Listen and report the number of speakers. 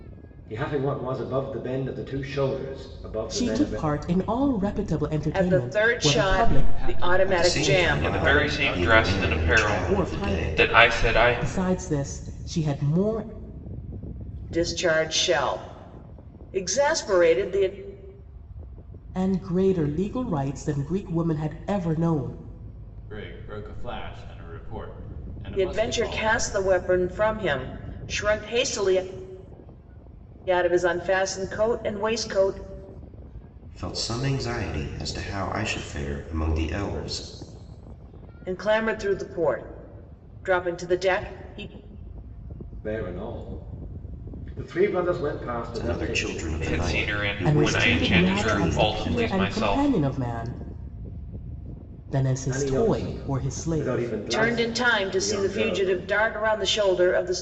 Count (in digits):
6